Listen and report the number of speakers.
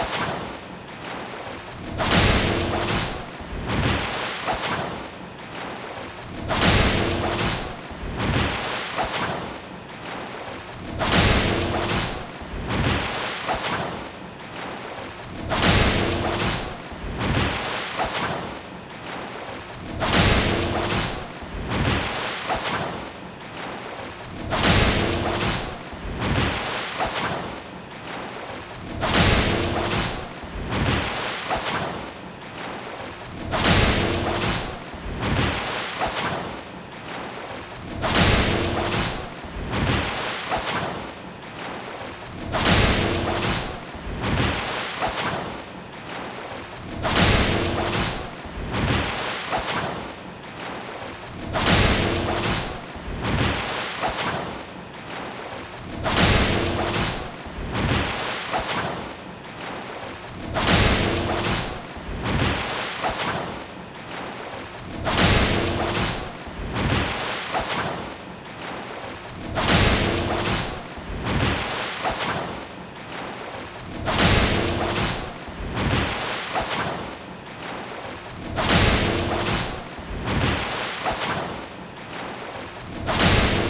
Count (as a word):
zero